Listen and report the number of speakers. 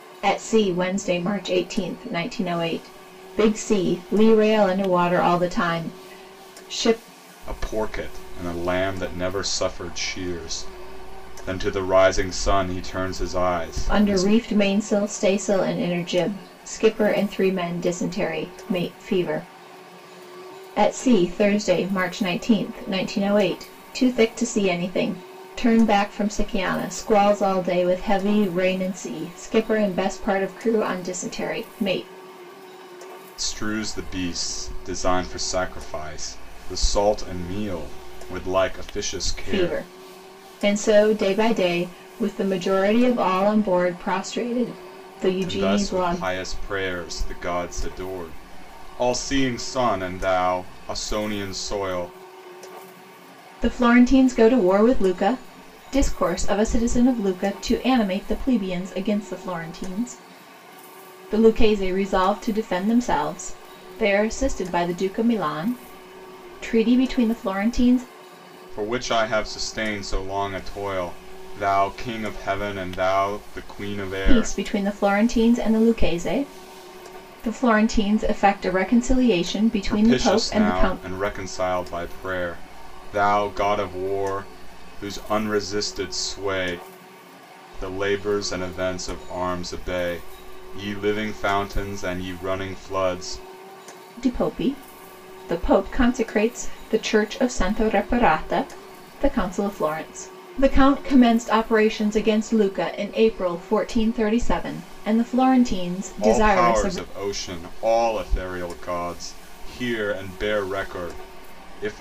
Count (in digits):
2